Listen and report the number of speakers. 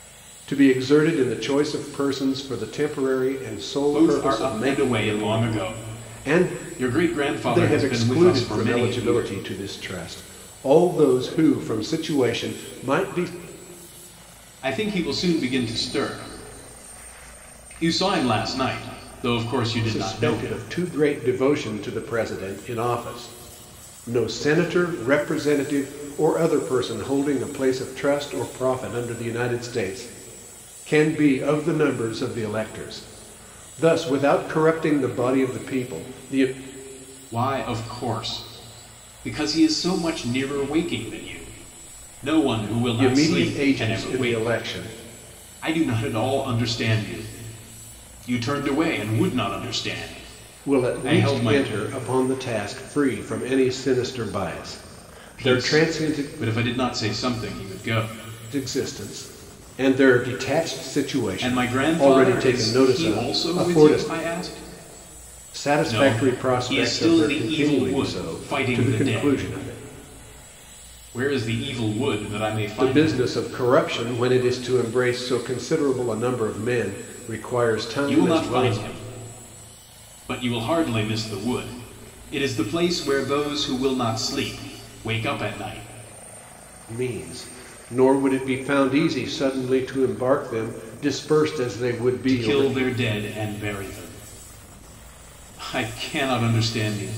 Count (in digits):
2